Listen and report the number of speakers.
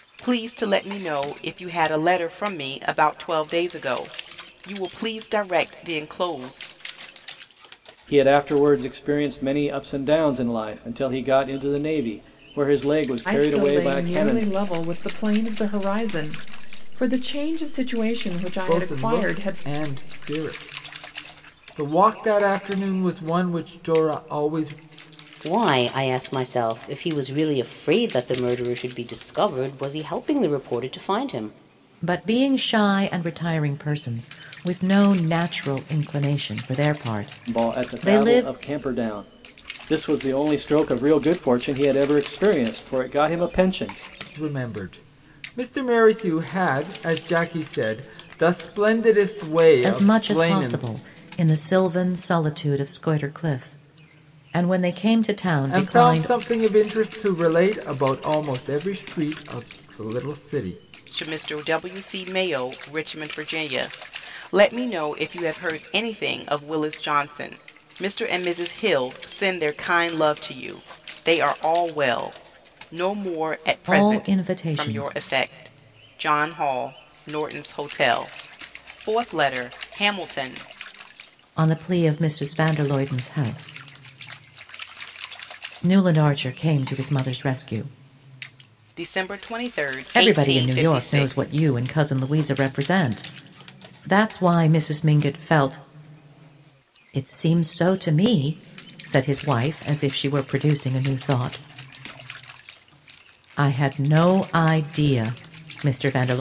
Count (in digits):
6